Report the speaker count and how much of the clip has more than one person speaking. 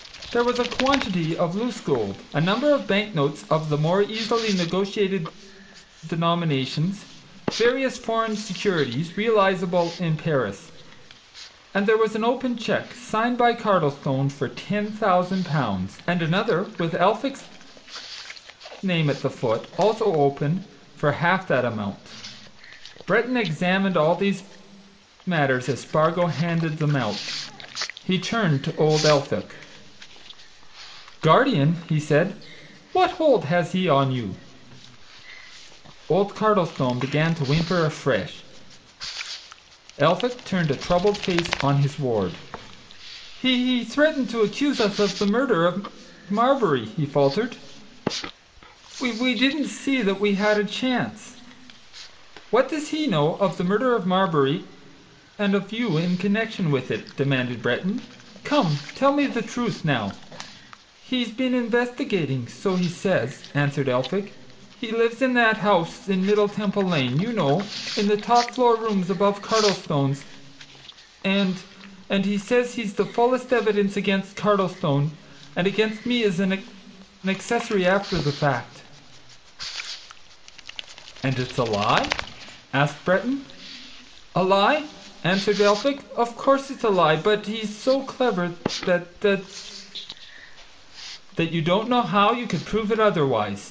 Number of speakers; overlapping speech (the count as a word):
one, no overlap